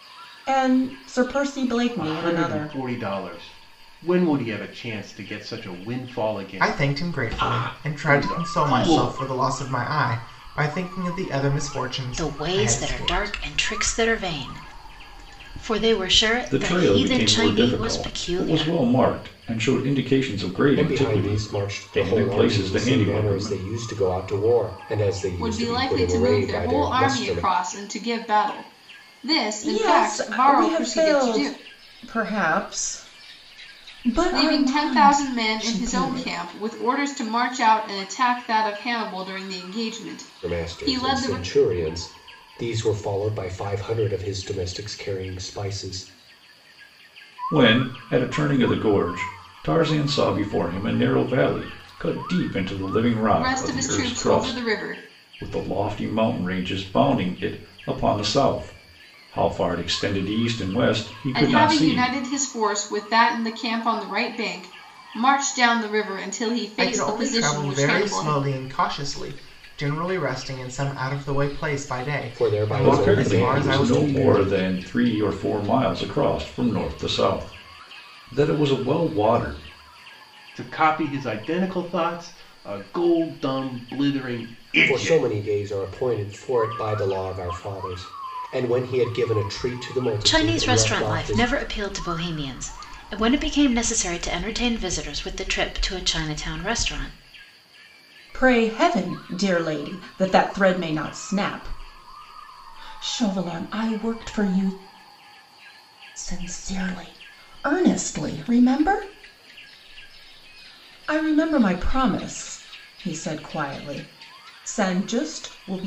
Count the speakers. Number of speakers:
seven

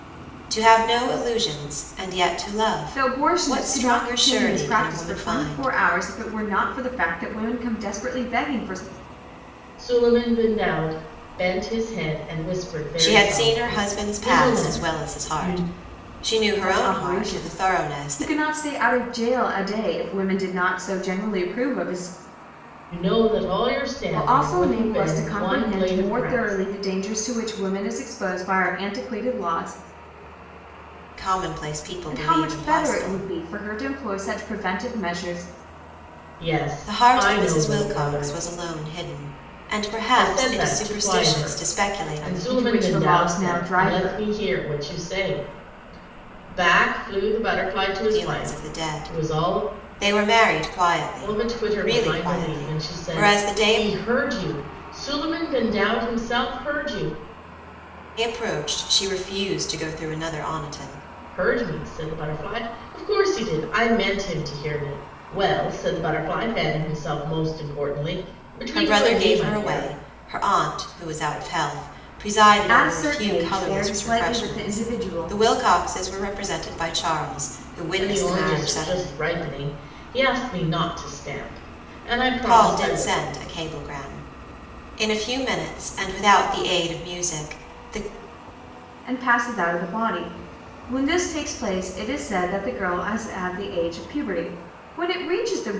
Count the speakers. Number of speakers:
three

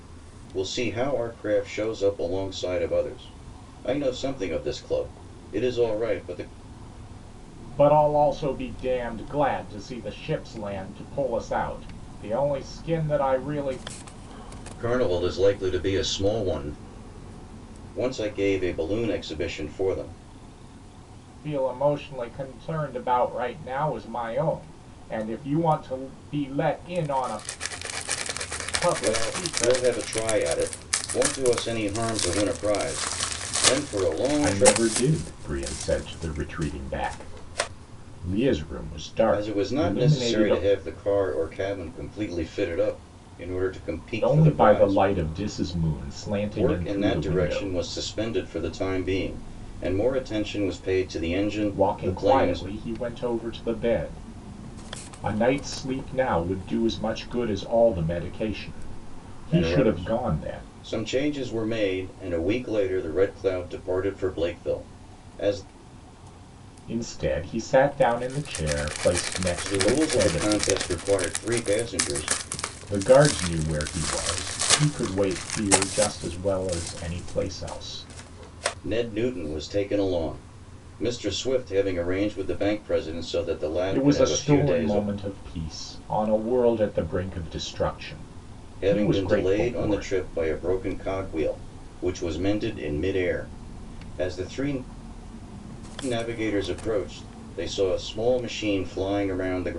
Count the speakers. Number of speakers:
two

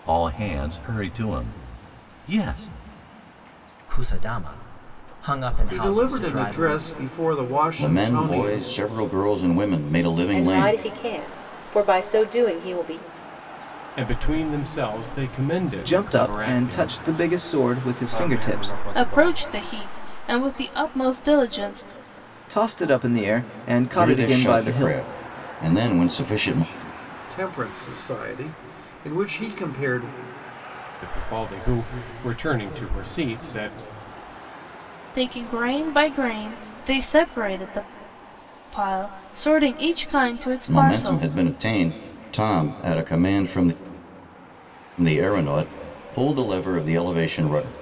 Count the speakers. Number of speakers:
nine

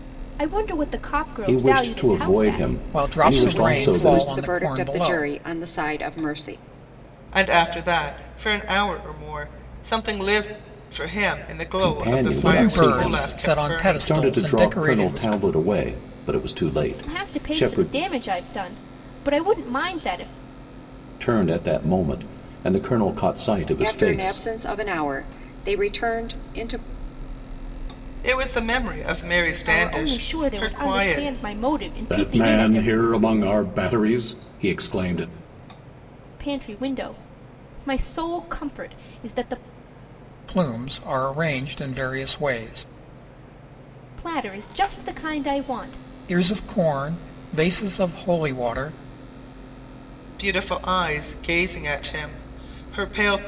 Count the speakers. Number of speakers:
five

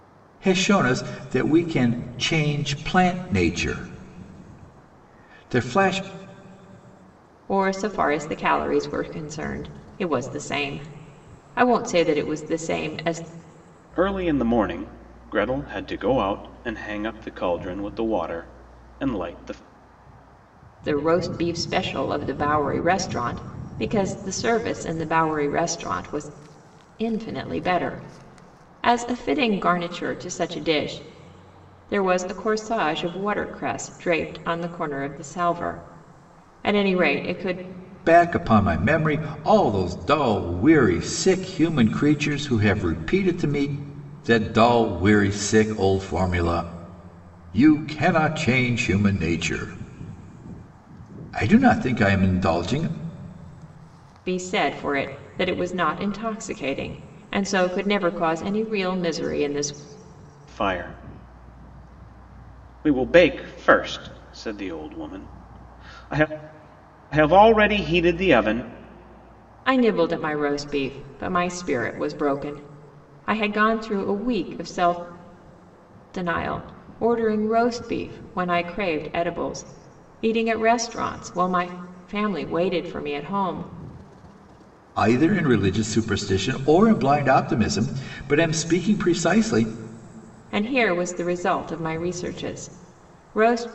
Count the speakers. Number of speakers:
three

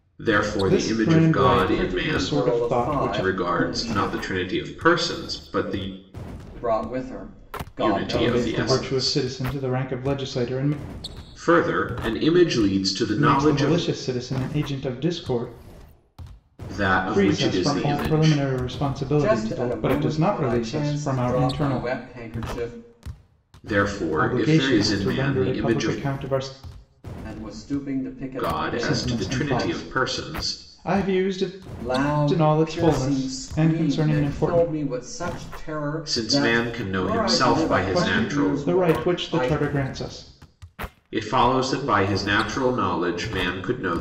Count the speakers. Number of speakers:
three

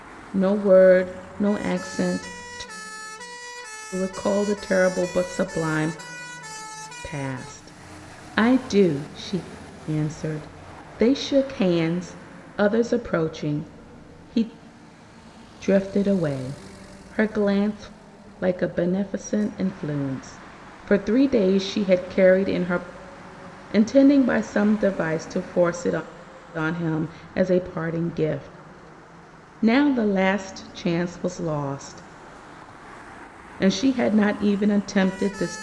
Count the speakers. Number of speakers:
one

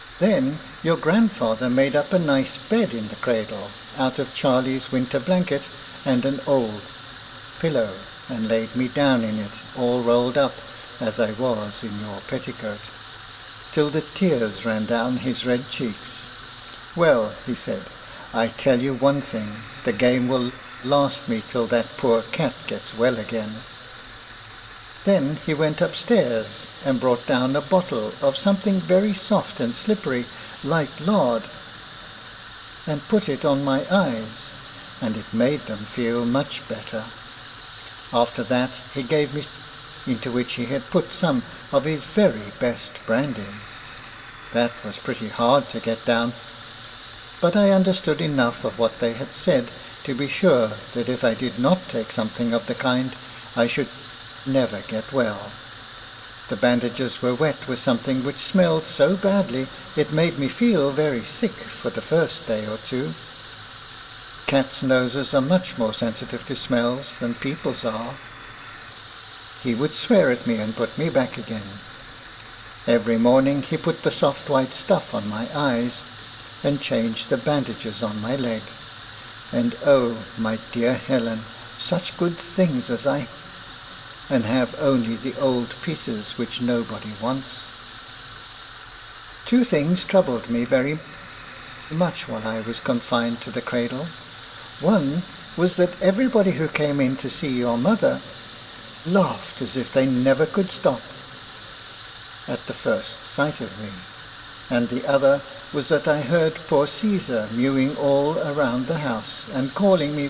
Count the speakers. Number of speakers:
one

